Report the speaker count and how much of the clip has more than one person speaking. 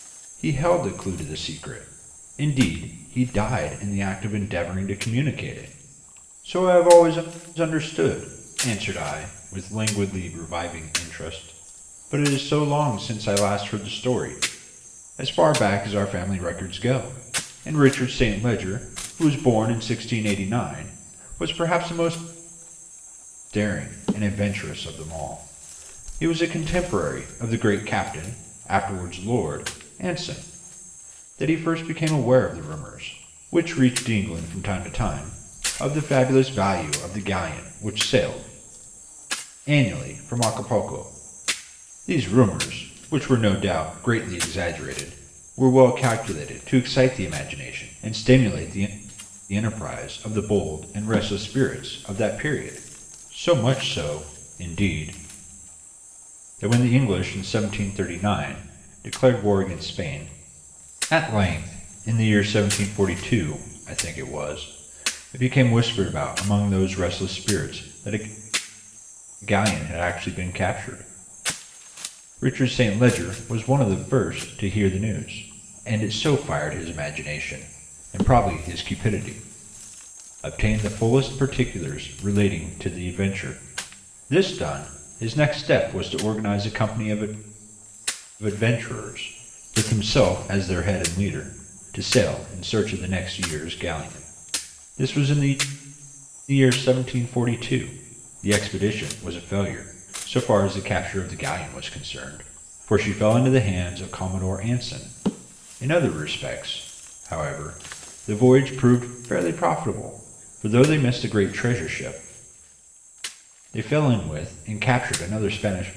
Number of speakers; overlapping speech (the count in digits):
1, no overlap